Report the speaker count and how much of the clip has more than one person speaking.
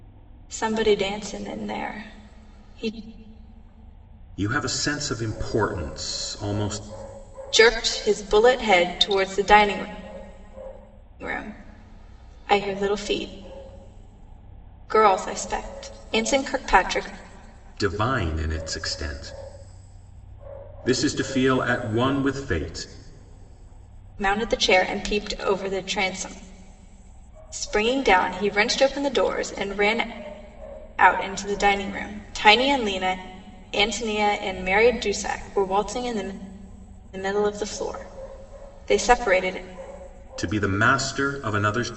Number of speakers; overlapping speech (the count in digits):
2, no overlap